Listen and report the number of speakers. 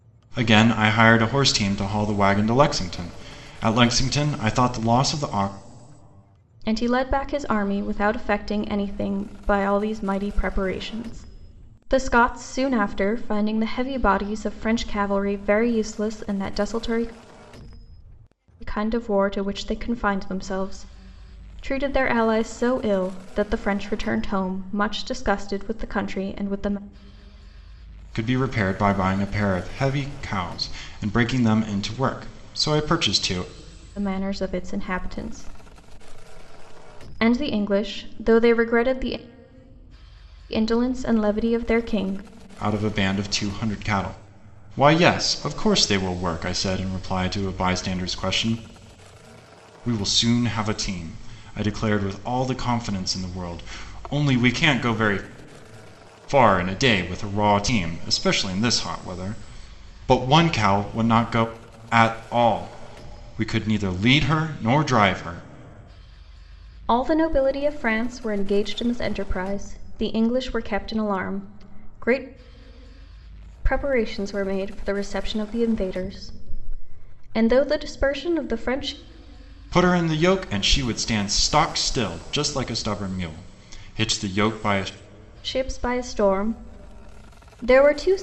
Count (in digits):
2